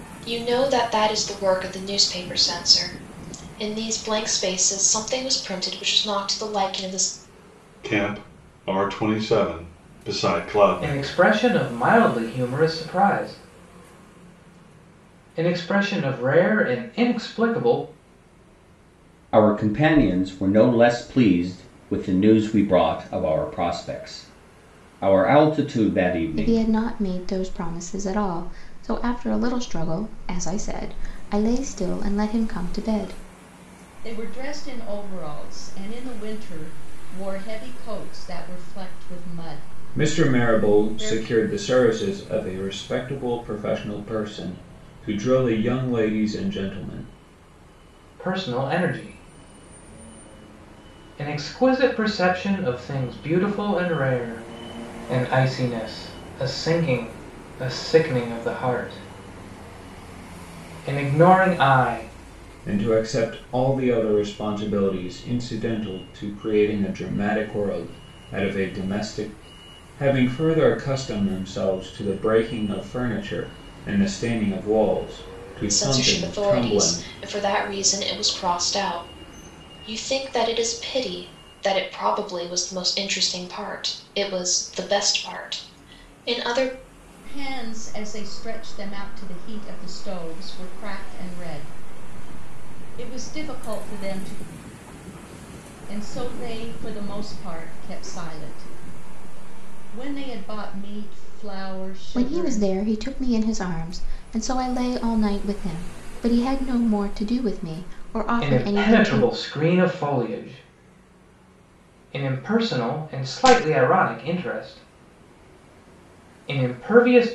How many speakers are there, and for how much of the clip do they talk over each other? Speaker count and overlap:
7, about 4%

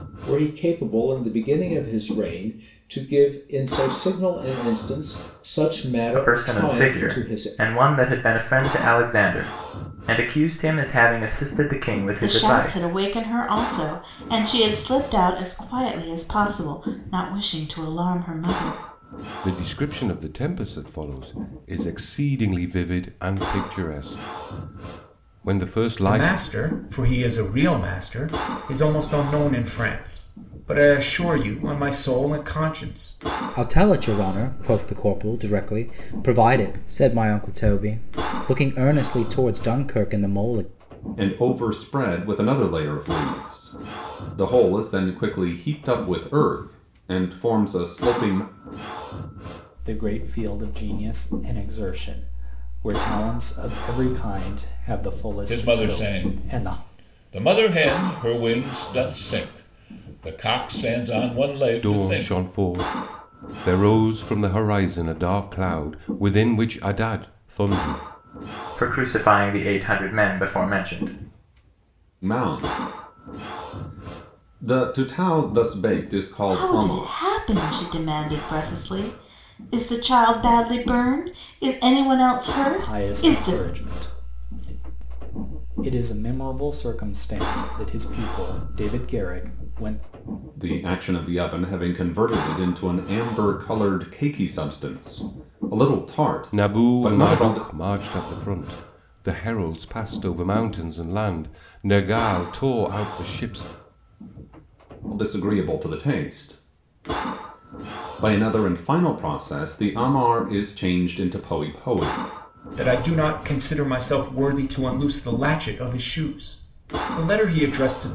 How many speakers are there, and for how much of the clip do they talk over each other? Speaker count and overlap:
9, about 6%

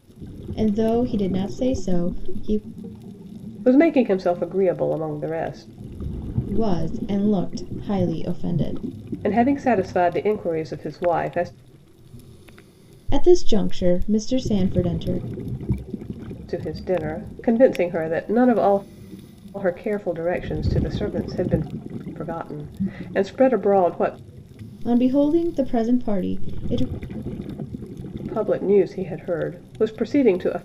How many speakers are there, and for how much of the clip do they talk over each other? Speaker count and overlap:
2, no overlap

